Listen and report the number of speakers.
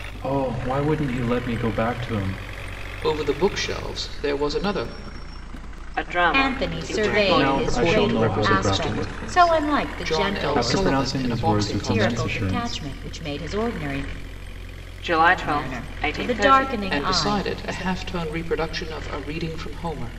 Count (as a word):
four